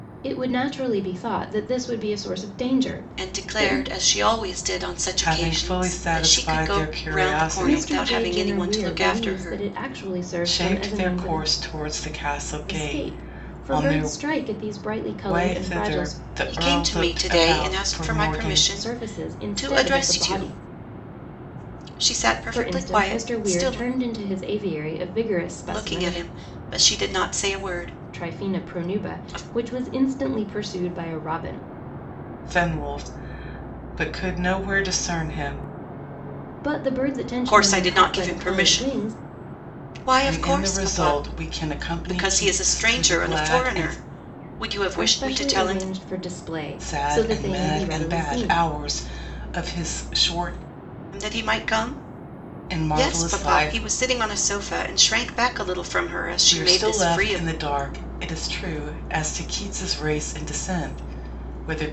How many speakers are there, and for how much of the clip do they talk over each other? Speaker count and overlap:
three, about 41%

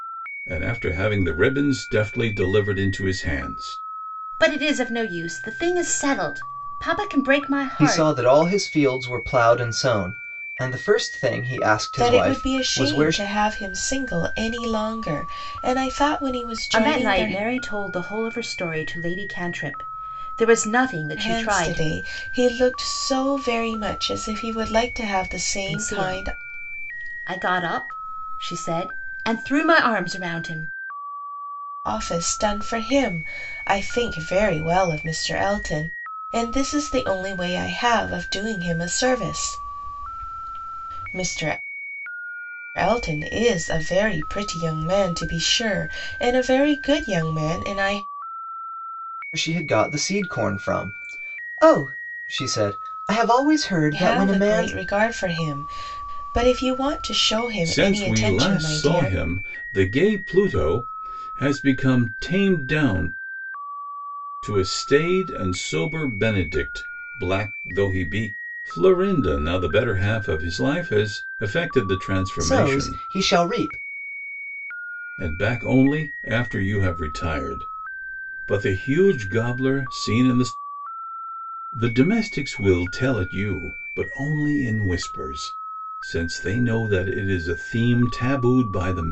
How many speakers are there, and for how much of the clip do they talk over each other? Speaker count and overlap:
four, about 8%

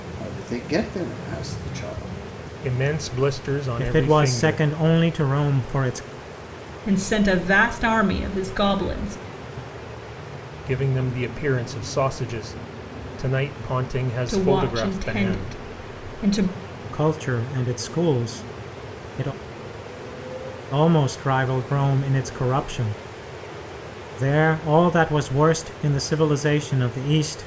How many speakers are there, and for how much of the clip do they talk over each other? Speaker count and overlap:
four, about 8%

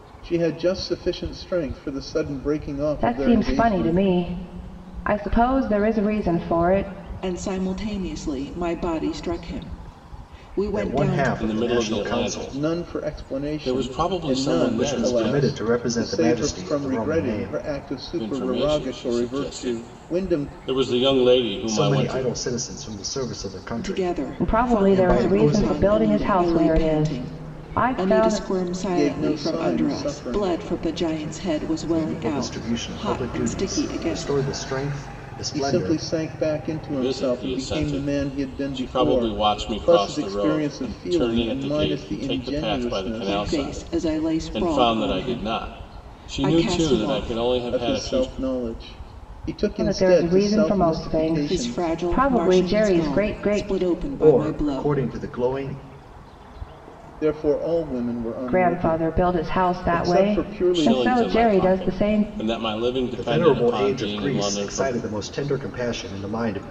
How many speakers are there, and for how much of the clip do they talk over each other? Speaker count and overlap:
five, about 61%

